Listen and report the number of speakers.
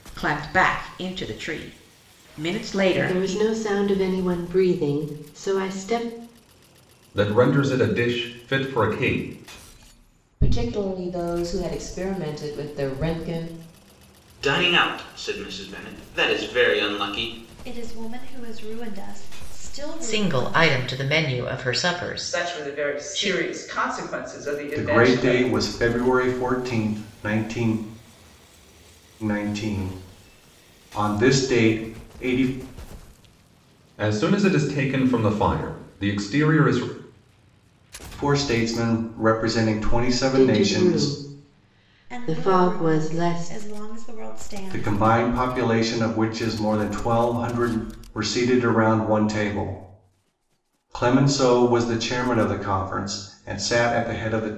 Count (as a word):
nine